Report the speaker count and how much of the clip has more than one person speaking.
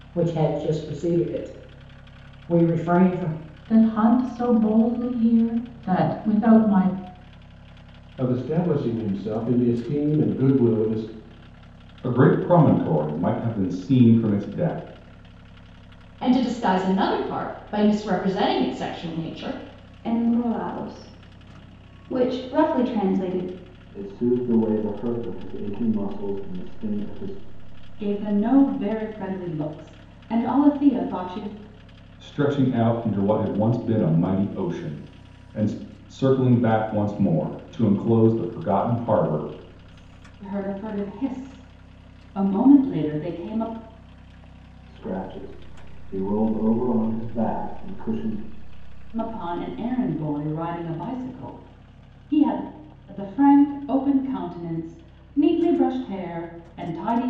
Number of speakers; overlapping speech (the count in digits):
8, no overlap